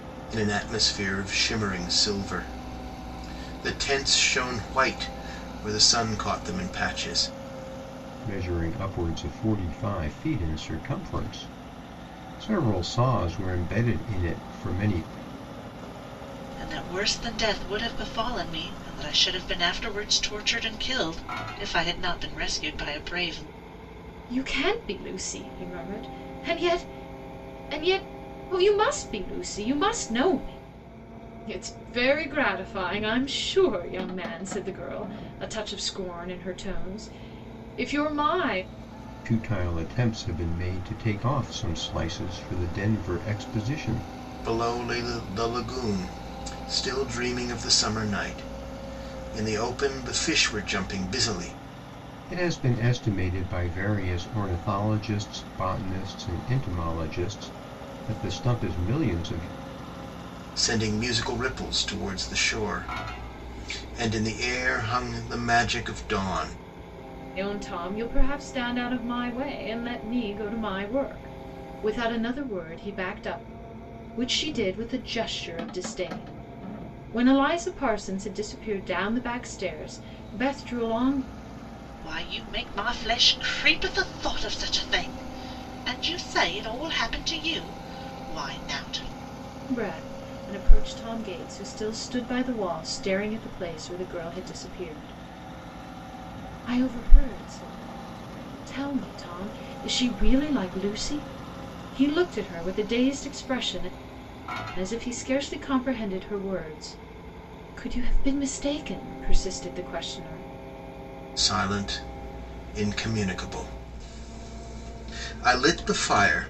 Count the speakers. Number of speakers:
4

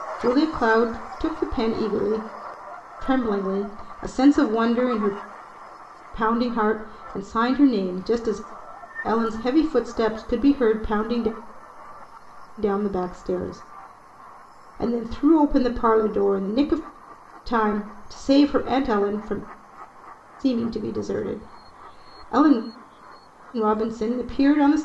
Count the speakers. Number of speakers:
1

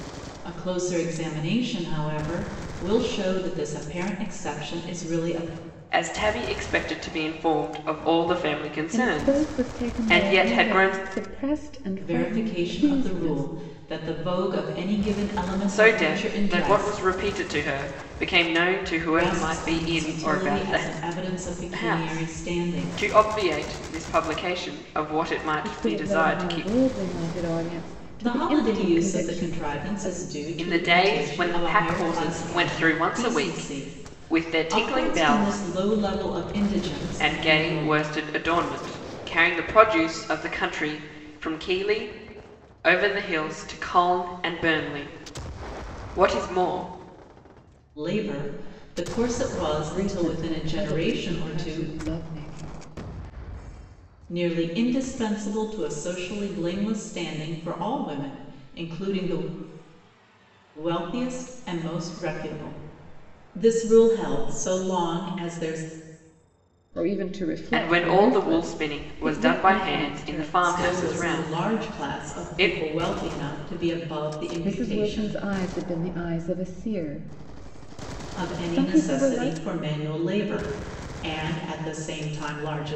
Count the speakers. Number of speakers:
3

